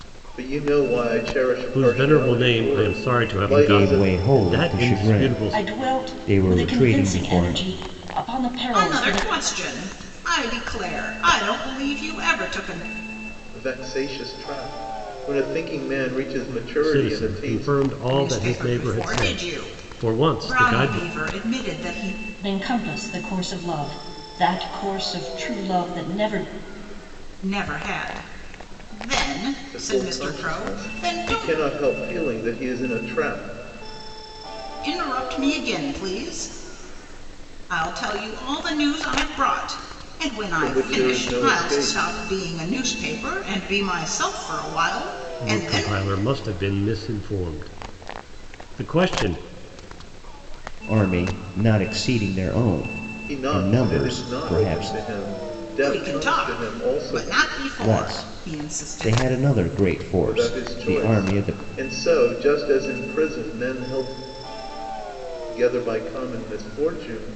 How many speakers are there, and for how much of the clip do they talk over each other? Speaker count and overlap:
five, about 30%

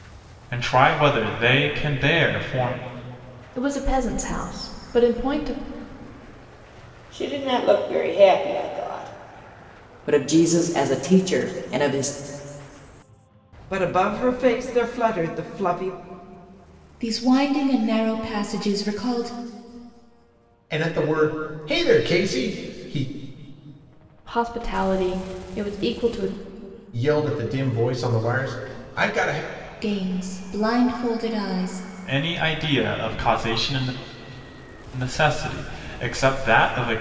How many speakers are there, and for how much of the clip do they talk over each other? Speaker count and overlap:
seven, no overlap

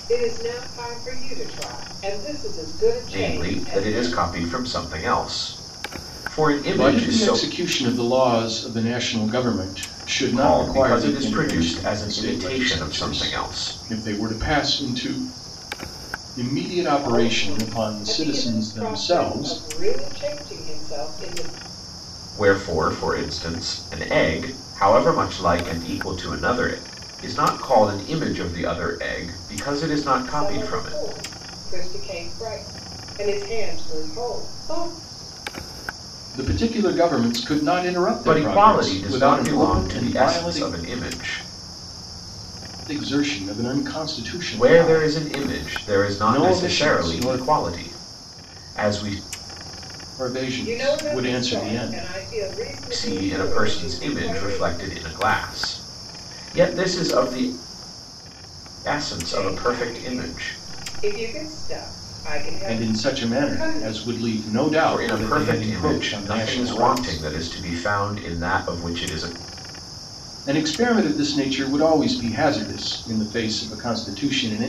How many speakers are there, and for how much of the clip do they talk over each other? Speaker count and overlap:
three, about 30%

